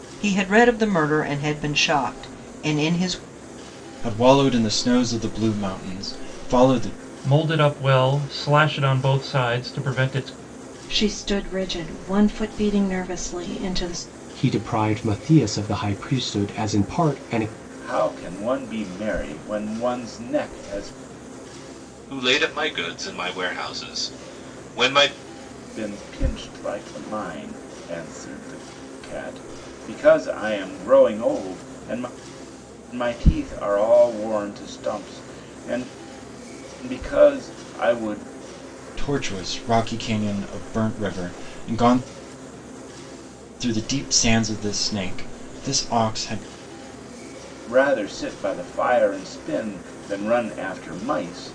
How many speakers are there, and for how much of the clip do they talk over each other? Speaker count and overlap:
7, no overlap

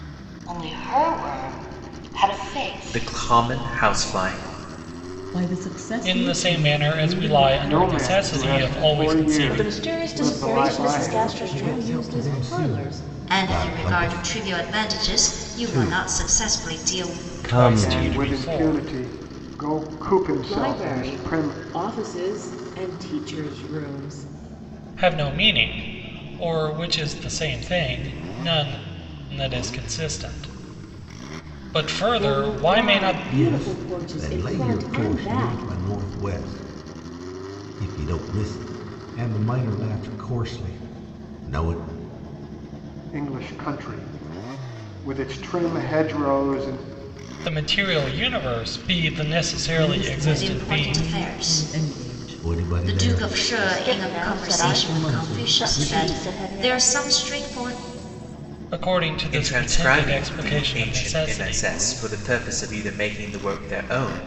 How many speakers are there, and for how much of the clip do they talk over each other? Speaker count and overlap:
10, about 41%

